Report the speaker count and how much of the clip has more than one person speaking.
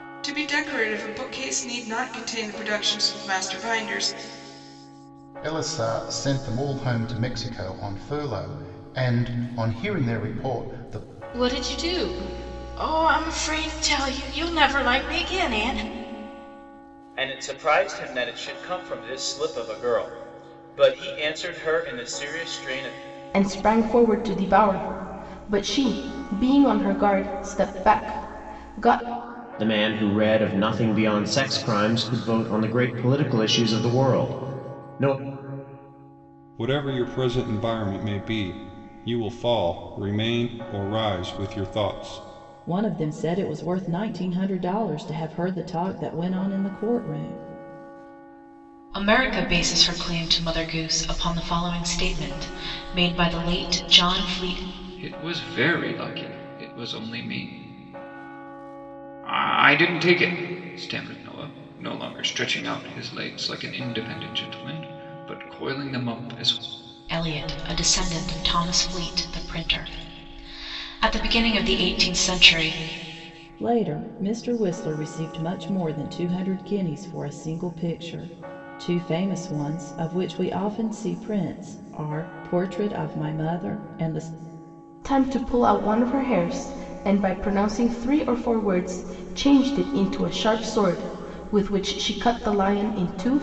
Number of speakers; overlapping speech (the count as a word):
ten, no overlap